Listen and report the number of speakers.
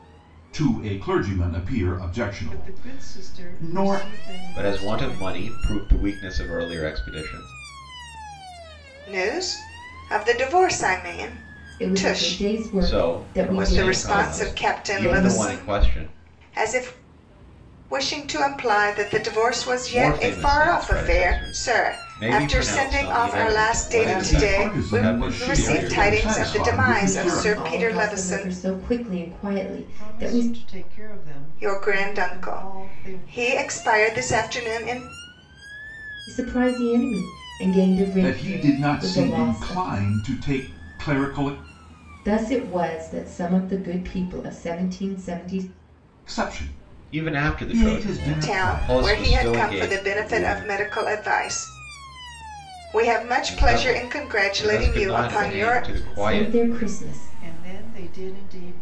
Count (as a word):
five